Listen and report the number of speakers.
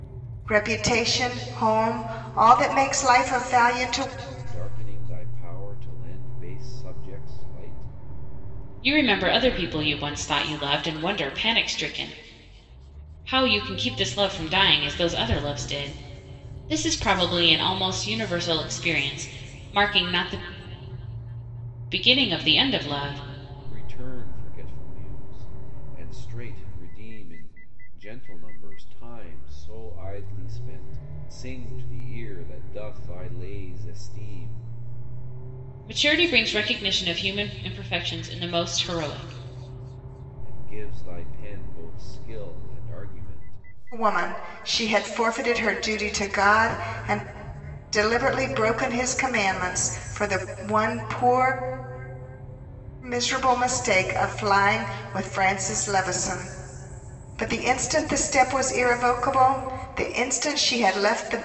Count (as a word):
three